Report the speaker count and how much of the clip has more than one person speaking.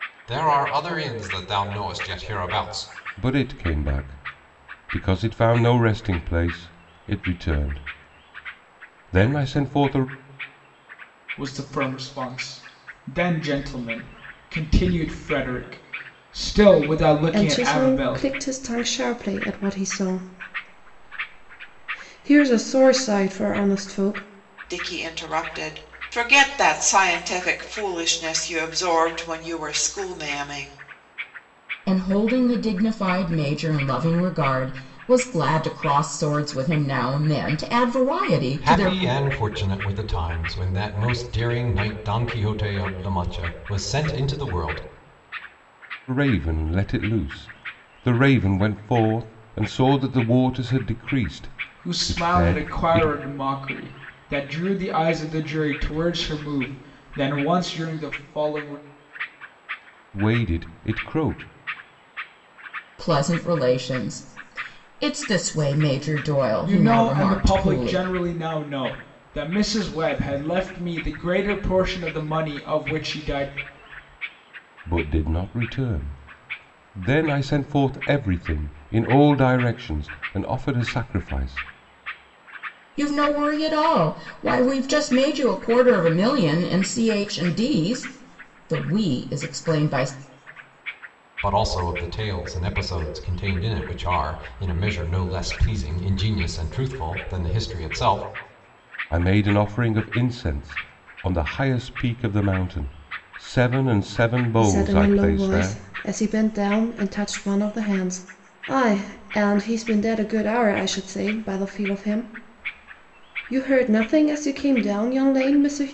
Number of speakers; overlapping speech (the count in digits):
6, about 5%